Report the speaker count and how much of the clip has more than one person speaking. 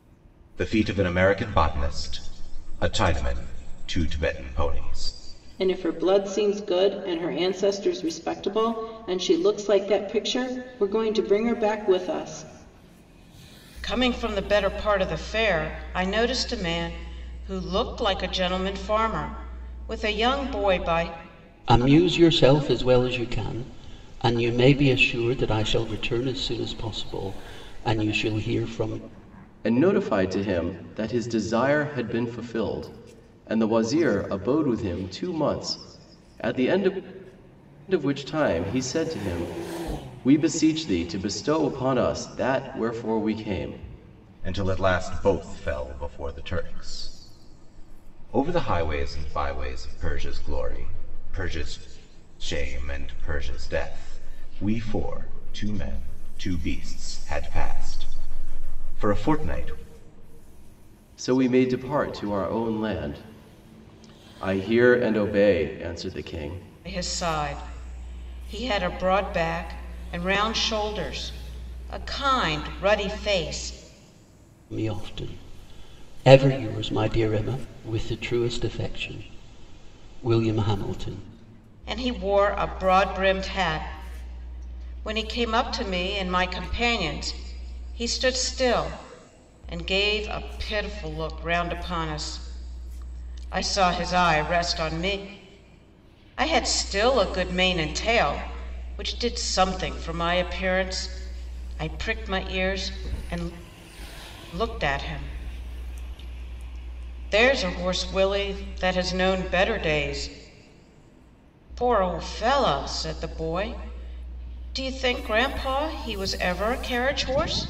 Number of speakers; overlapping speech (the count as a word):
five, no overlap